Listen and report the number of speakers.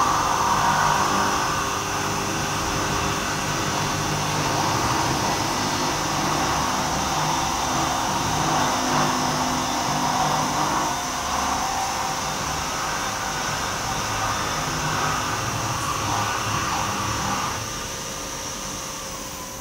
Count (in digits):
0